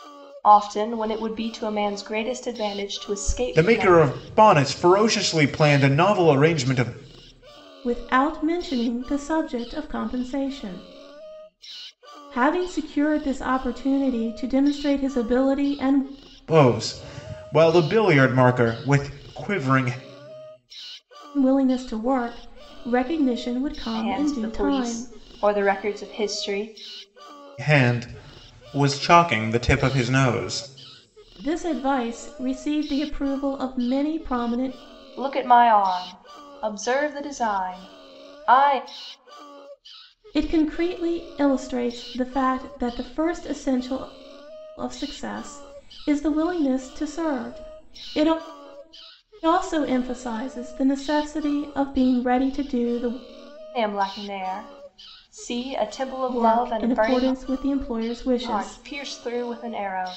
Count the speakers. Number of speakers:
3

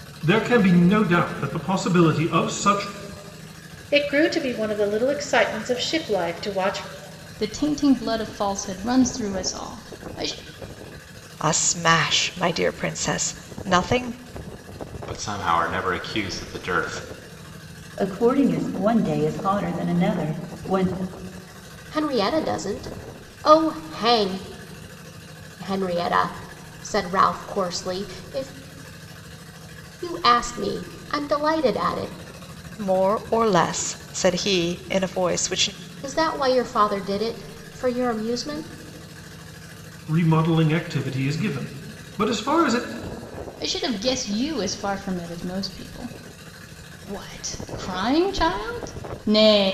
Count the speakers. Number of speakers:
7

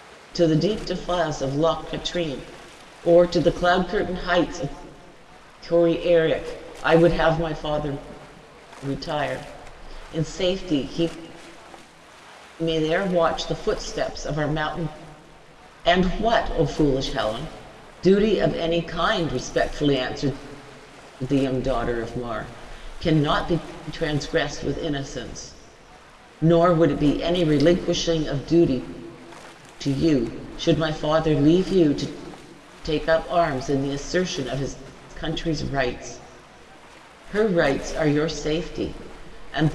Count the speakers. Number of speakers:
1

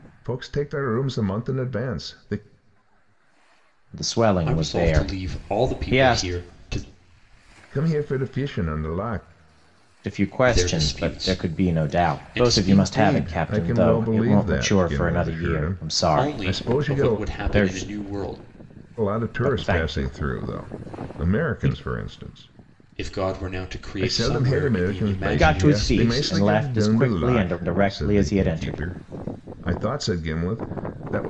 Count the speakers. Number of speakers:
3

